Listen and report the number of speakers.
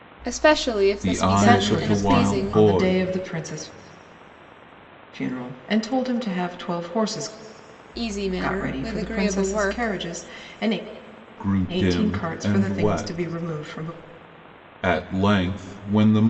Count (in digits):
3